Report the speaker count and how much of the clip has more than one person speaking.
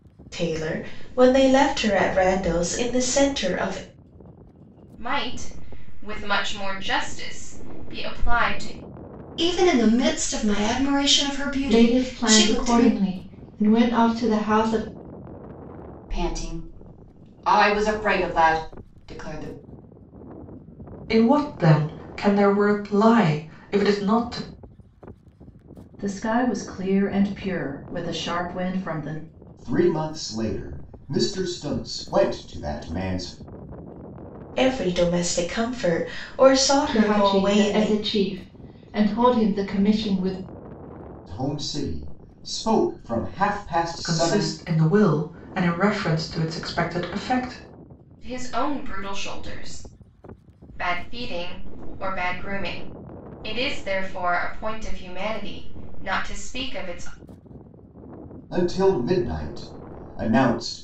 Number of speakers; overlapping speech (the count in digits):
8, about 5%